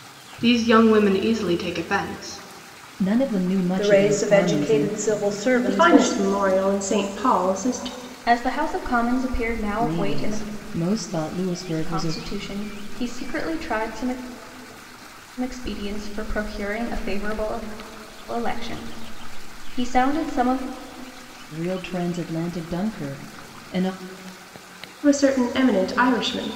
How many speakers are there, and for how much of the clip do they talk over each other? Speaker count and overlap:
five, about 11%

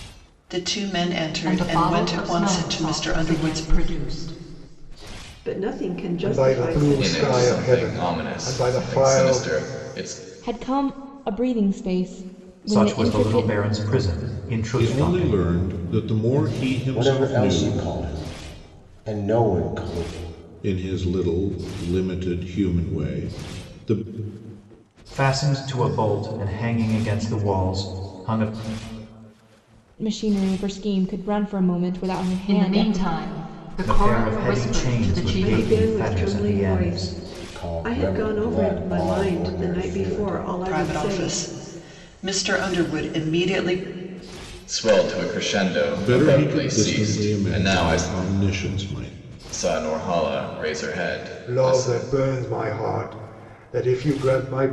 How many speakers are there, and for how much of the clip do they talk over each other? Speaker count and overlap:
nine, about 34%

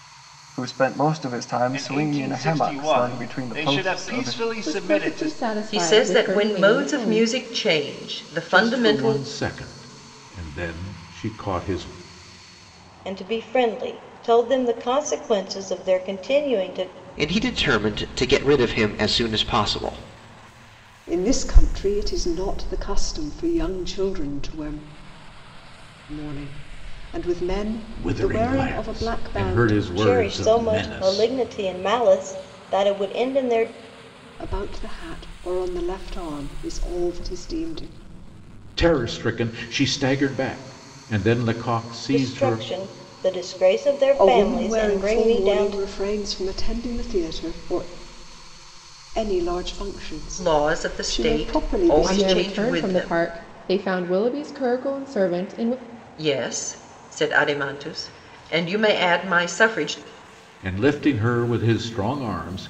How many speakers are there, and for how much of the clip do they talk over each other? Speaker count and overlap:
eight, about 23%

